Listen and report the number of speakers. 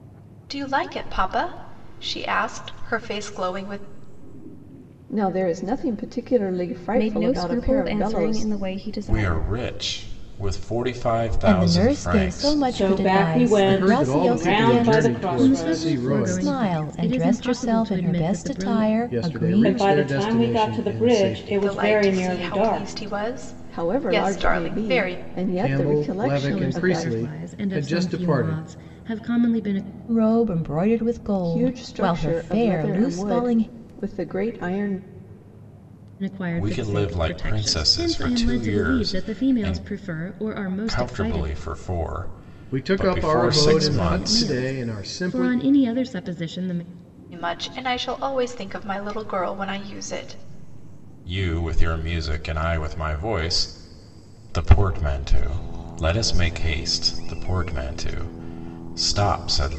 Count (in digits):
8